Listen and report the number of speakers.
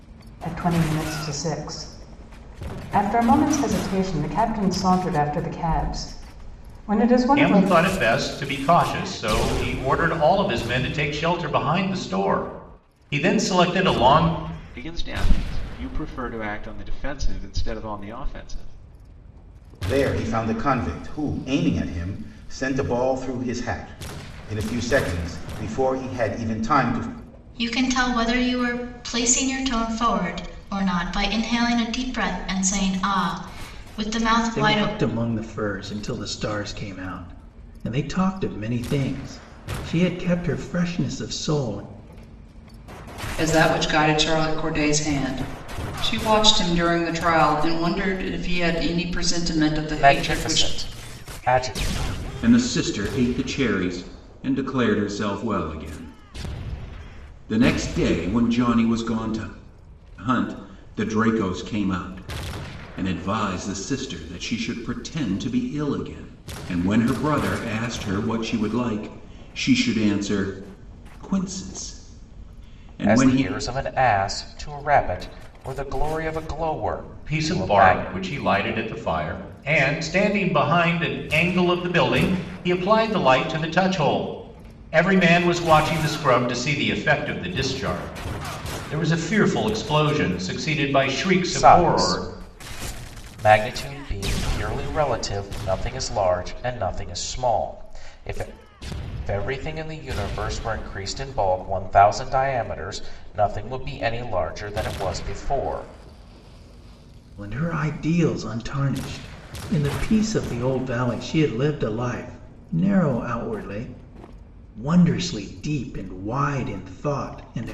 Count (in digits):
9